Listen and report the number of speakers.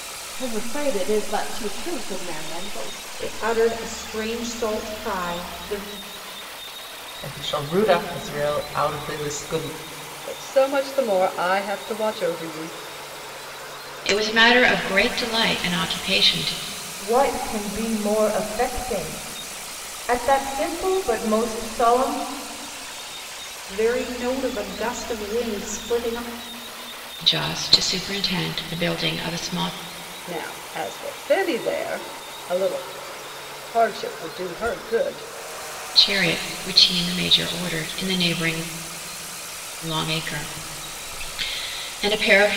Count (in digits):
6